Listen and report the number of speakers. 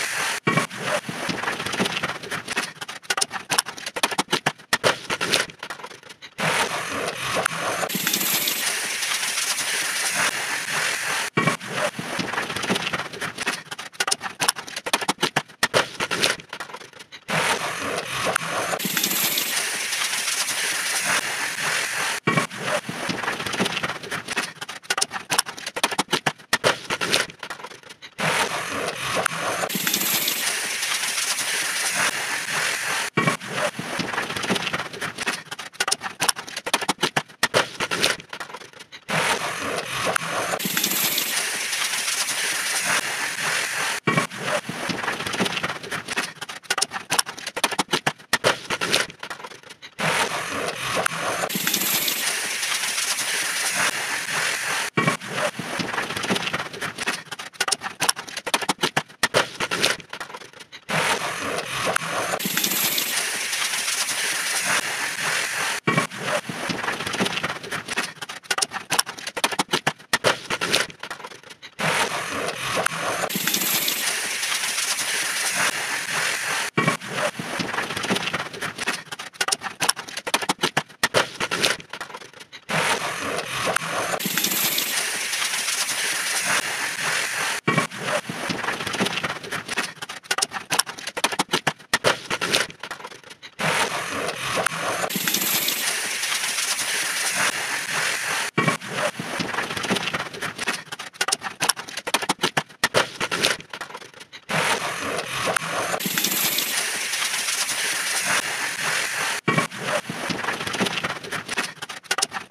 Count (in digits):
0